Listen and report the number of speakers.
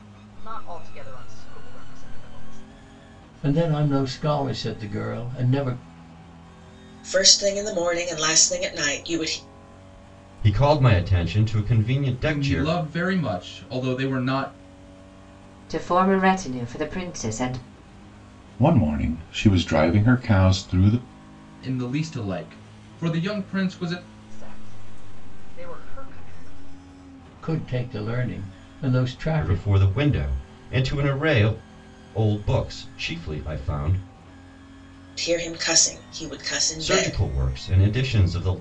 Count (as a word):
seven